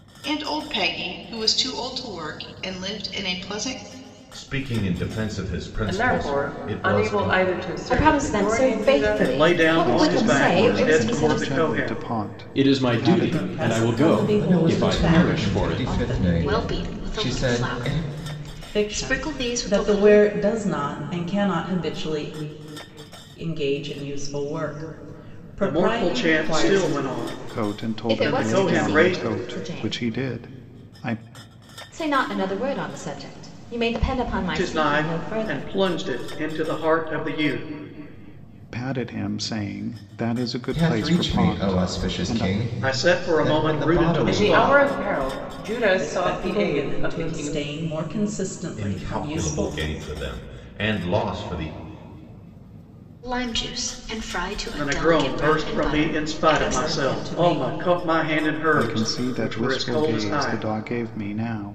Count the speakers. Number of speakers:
ten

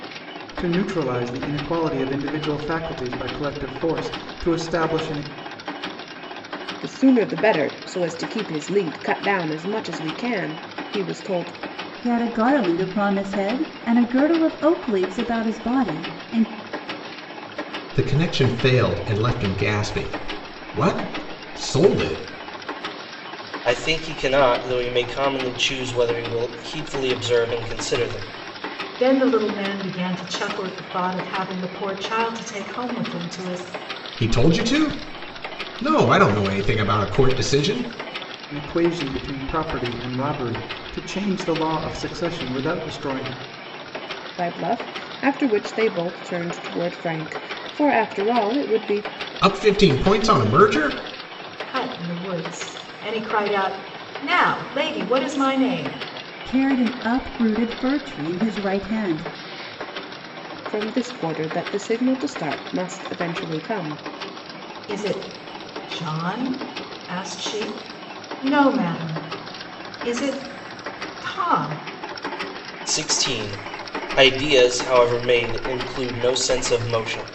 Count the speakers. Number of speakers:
six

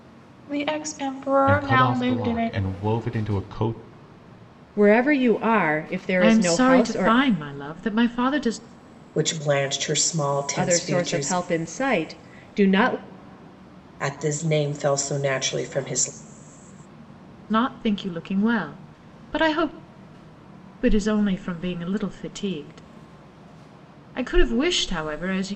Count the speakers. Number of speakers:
five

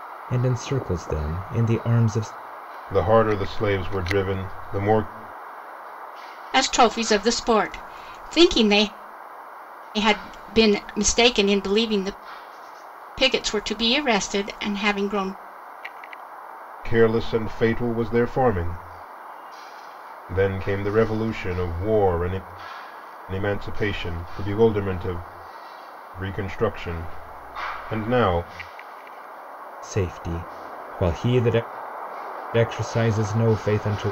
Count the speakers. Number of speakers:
three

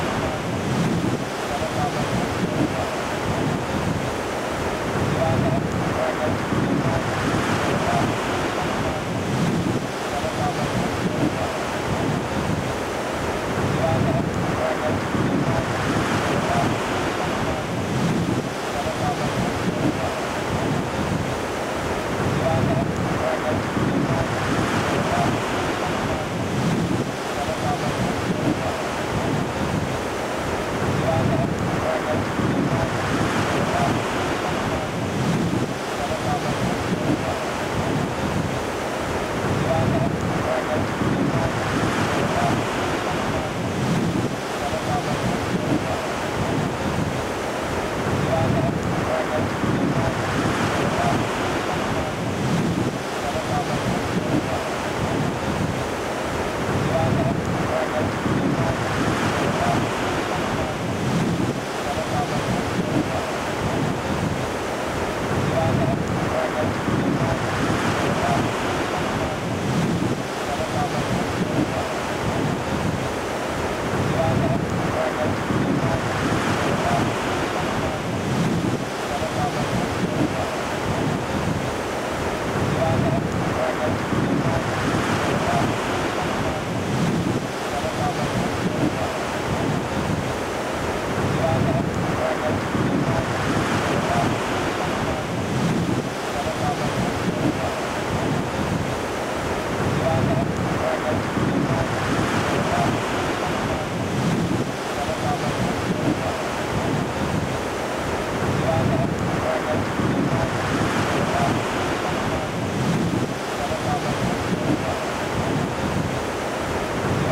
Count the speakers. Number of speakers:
zero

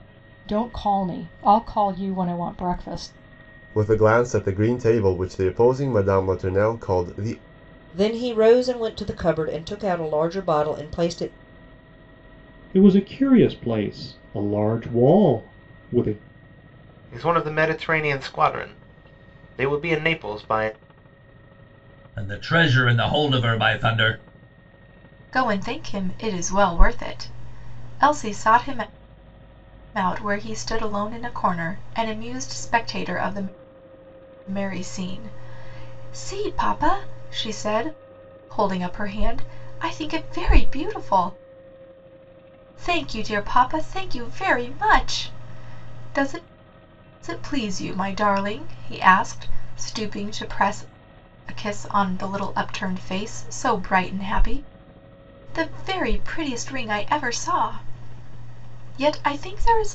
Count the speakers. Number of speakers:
seven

